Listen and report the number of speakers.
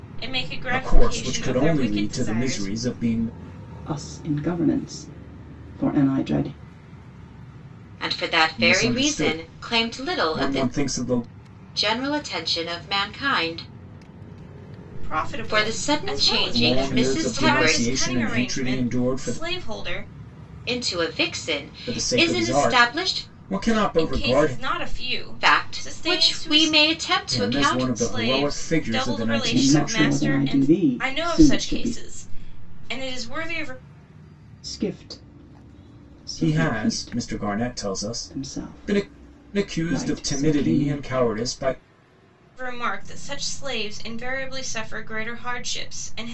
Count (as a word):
four